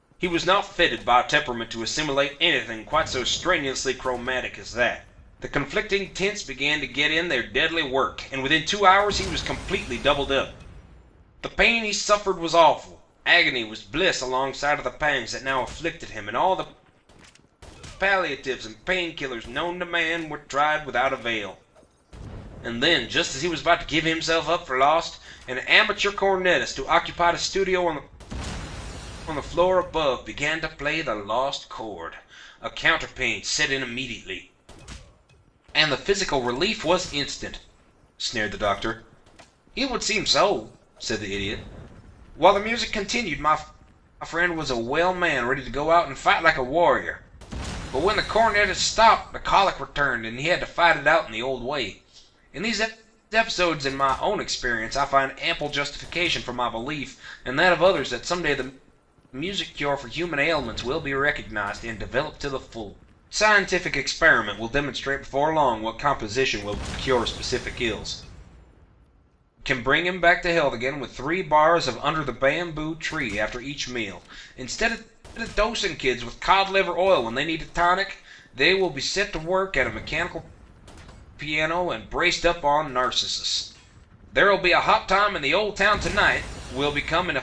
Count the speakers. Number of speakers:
one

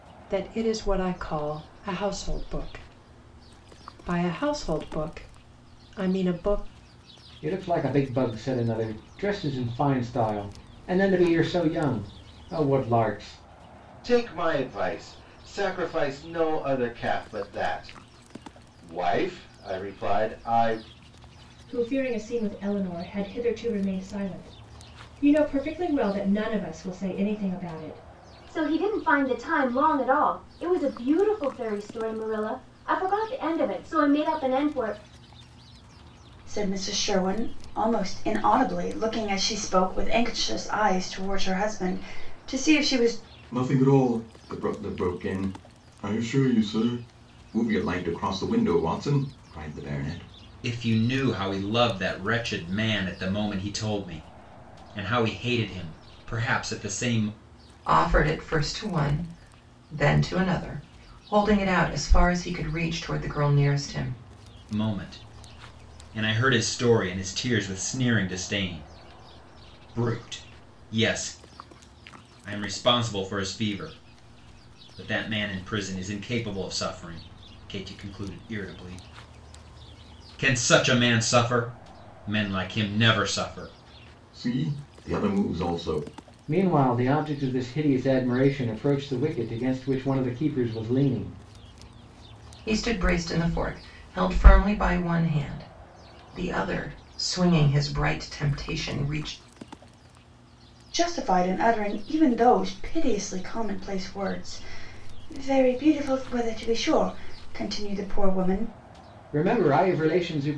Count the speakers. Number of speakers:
nine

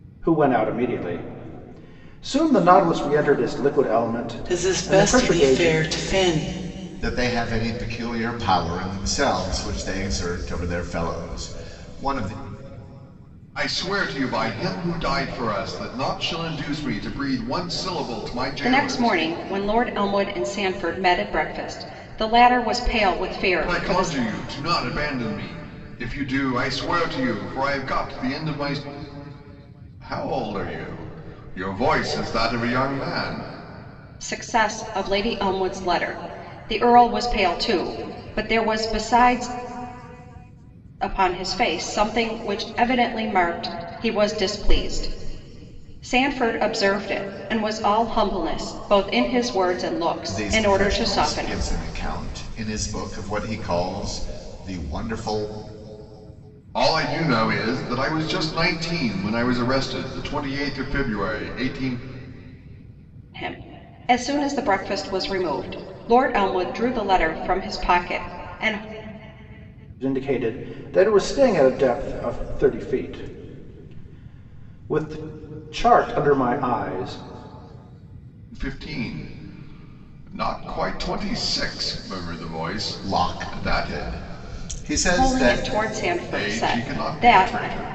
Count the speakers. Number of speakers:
five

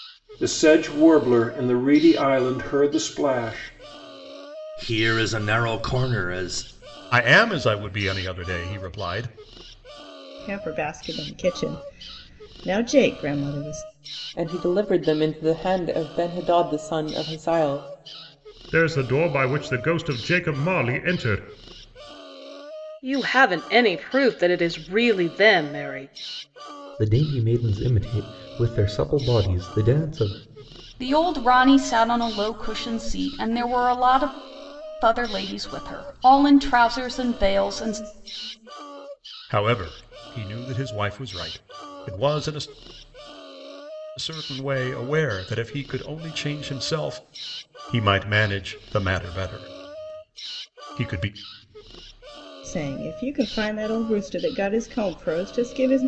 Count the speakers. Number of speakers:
nine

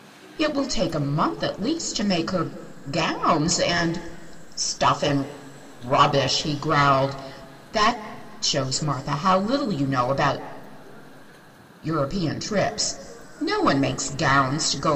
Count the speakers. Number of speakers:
one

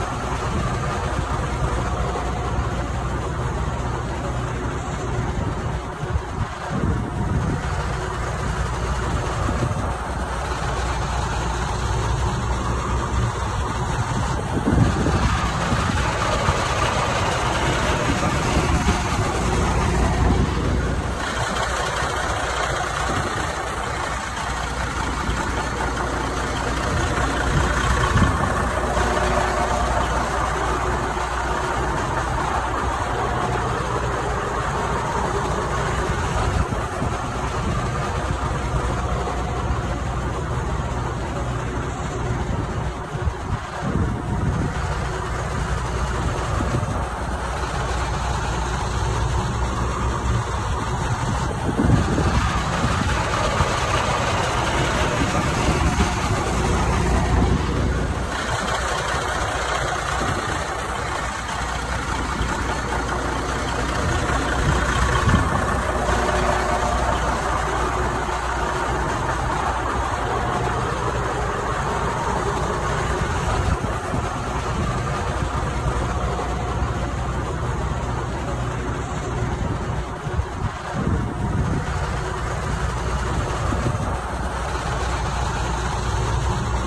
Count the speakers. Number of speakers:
zero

